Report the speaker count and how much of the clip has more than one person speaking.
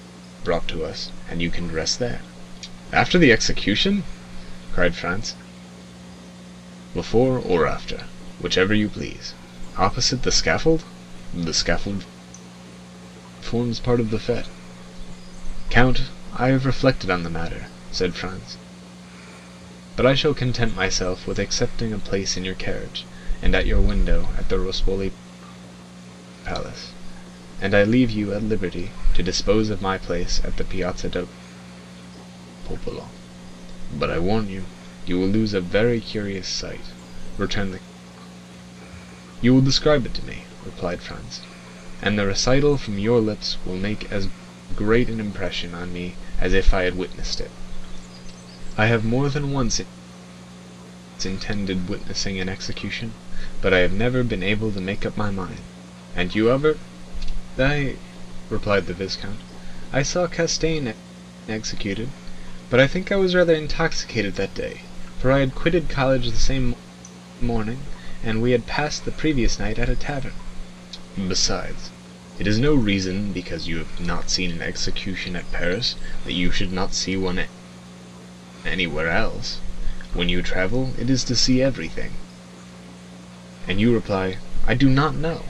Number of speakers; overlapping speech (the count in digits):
1, no overlap